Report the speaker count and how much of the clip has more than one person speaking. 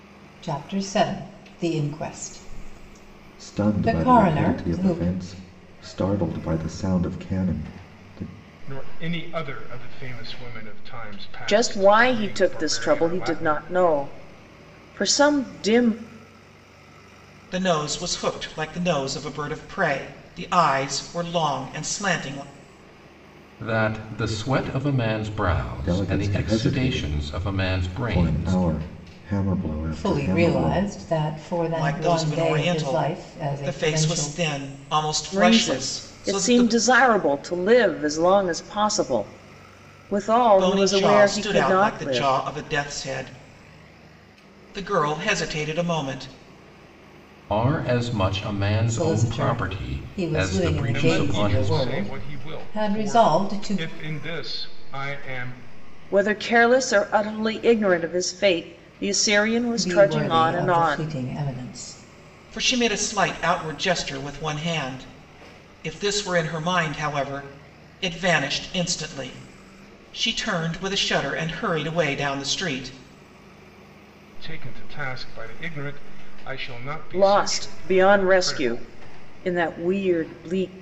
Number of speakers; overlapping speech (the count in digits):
6, about 27%